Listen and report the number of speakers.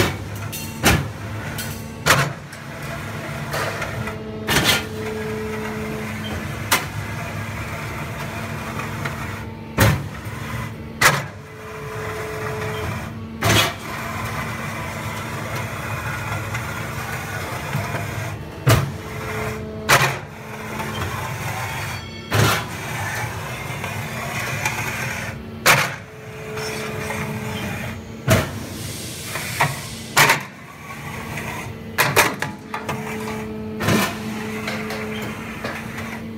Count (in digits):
0